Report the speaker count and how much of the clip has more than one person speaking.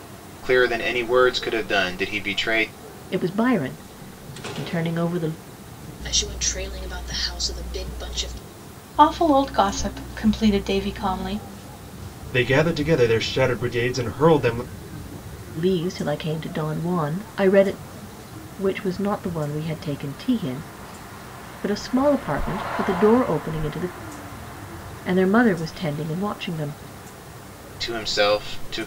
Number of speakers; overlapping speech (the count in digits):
5, no overlap